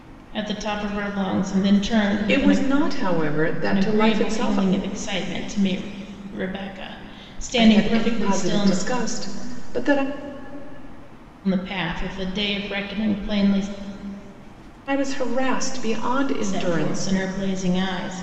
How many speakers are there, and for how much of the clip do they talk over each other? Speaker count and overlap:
two, about 18%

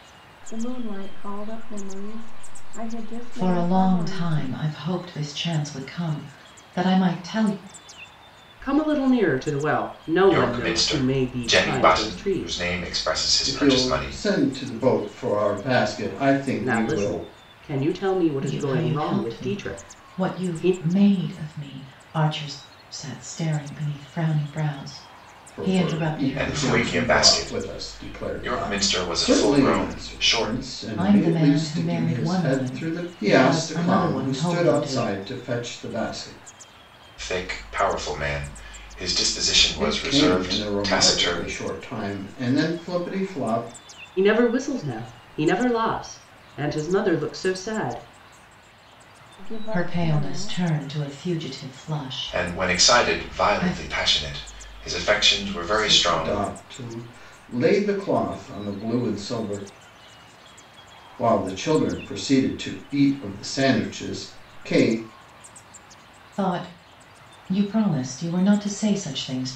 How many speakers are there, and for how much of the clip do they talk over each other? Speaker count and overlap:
five, about 30%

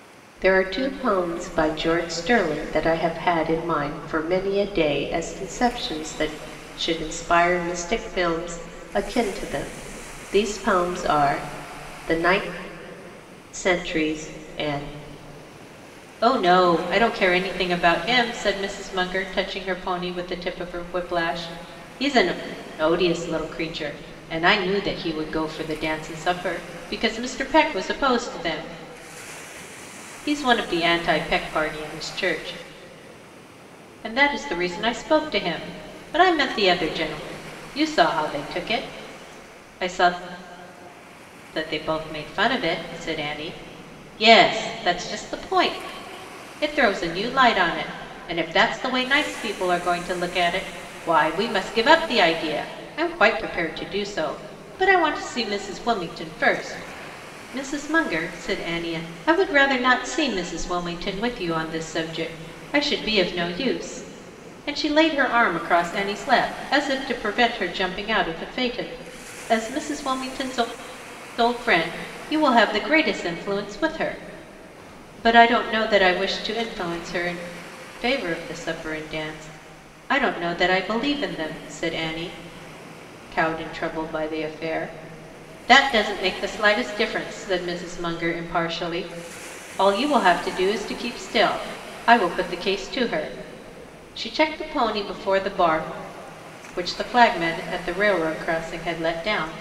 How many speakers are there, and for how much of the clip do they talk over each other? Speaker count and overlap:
one, no overlap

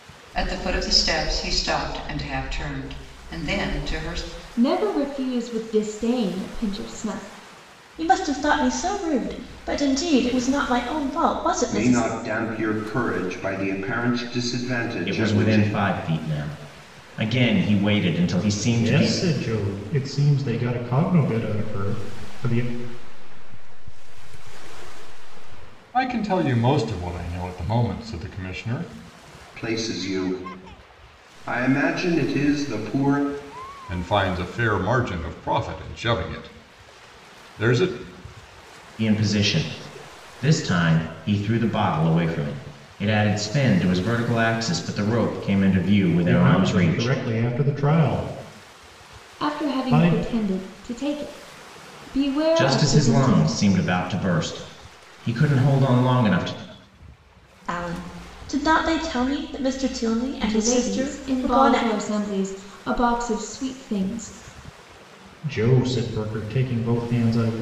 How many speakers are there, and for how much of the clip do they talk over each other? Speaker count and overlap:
eight, about 10%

